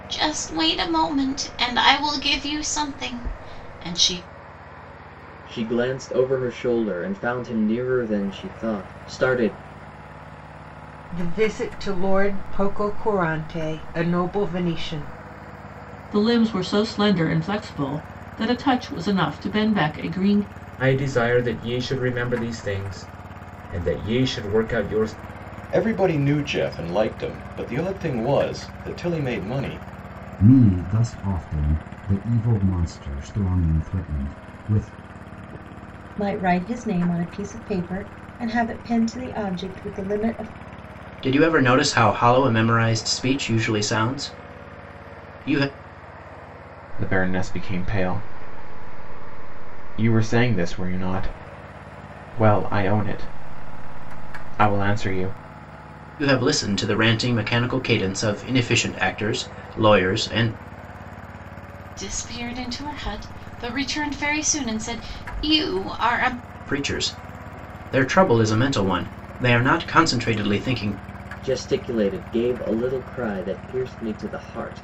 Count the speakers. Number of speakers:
10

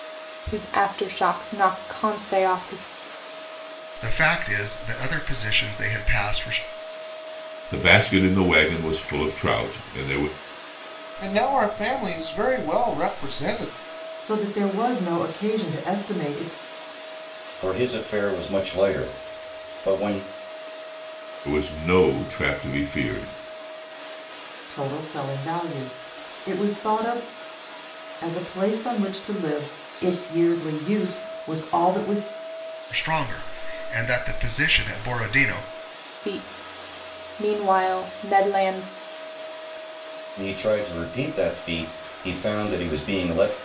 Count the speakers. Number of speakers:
6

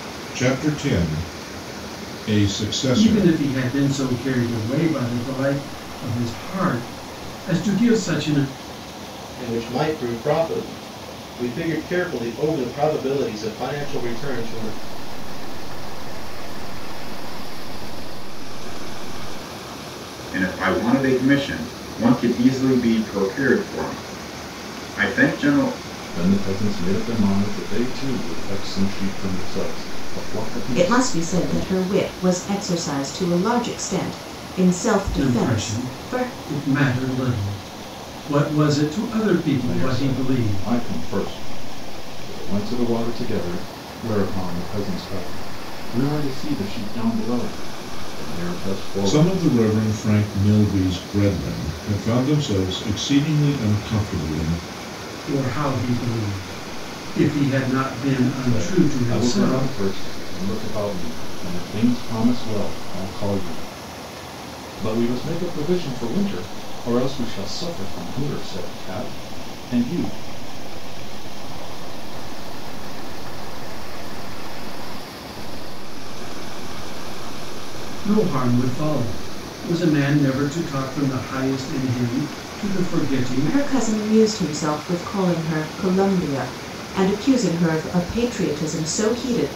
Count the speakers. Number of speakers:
7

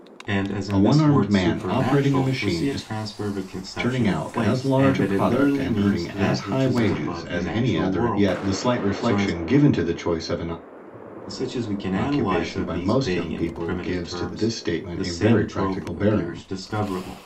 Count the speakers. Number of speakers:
2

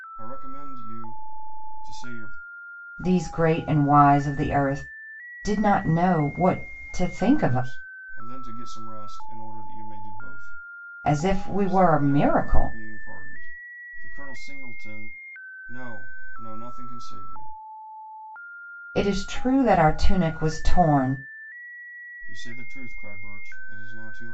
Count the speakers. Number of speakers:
2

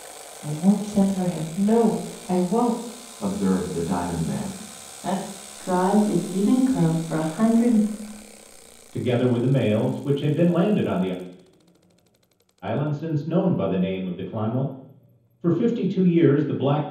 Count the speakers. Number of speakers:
4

